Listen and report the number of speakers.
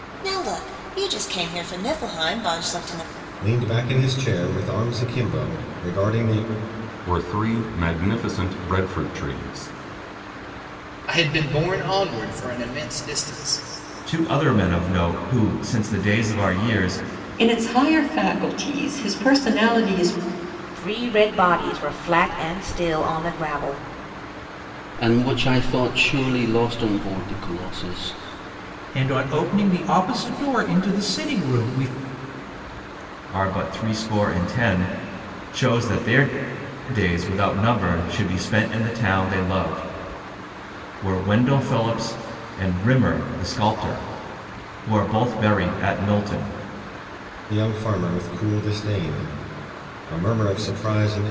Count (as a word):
nine